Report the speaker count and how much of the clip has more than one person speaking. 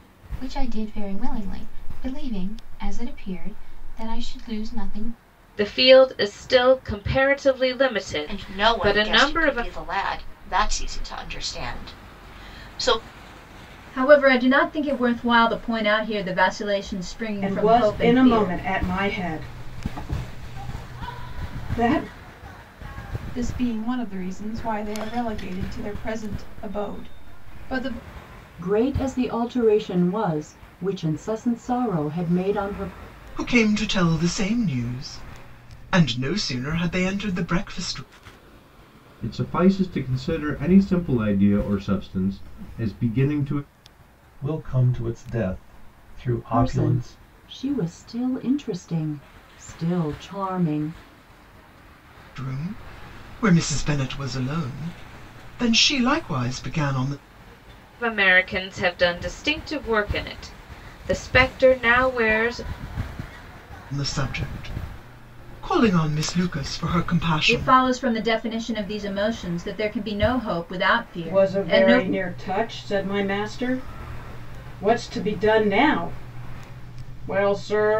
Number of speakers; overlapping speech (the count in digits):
10, about 6%